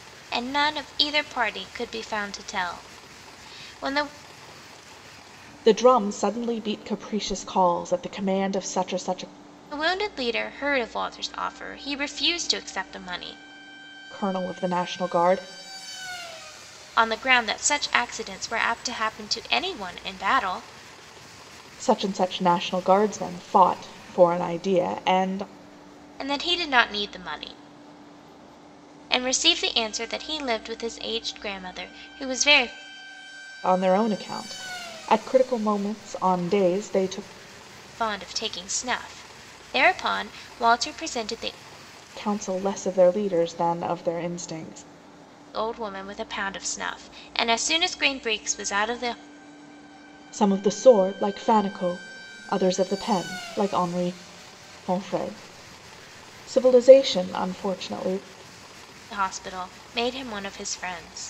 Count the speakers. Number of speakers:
two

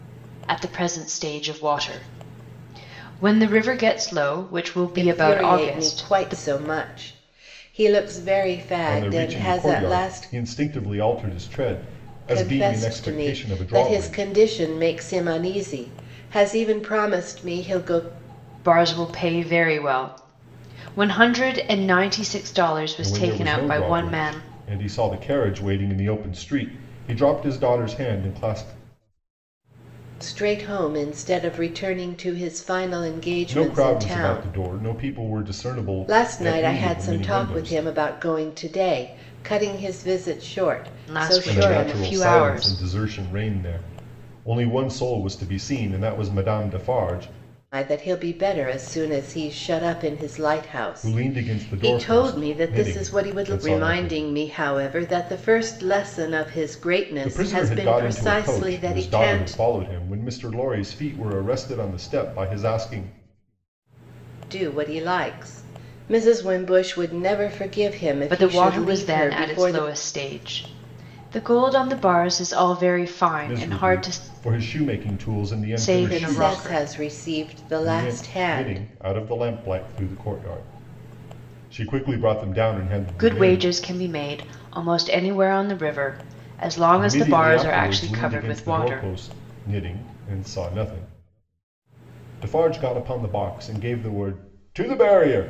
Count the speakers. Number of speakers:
three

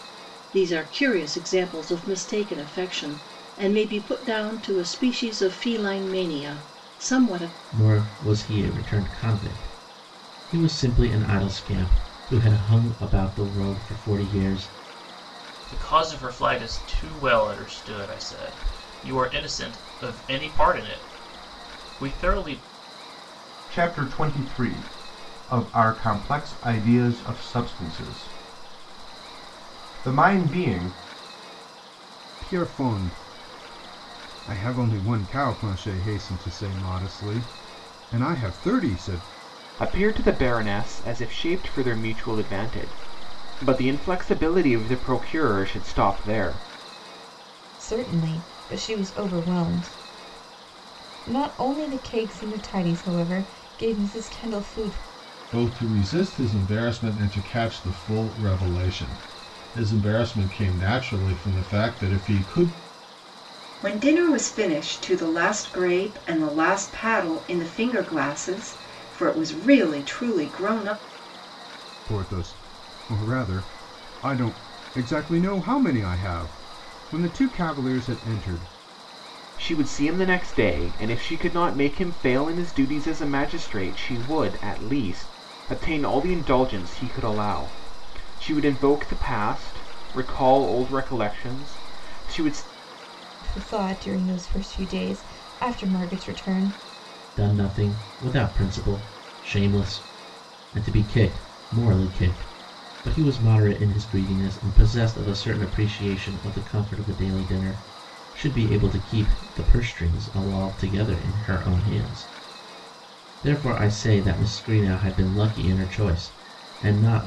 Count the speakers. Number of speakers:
nine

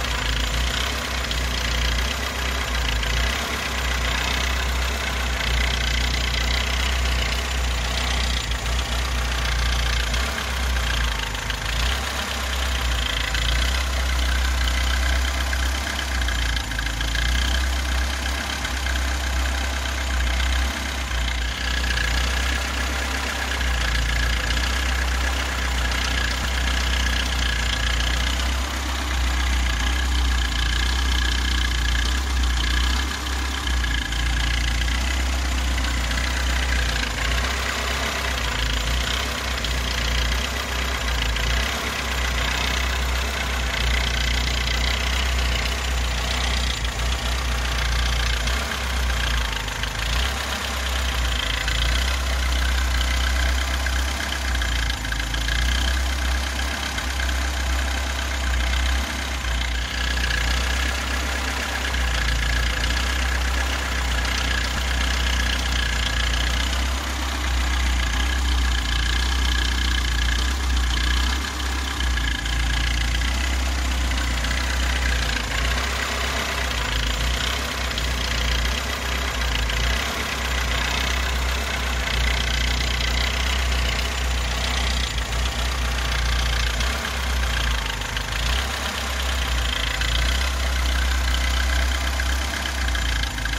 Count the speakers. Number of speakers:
zero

